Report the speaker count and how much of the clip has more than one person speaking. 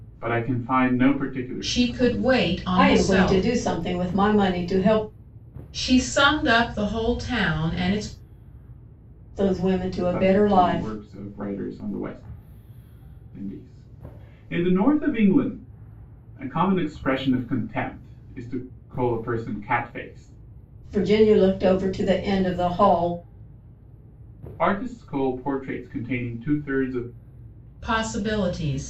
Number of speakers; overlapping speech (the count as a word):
three, about 8%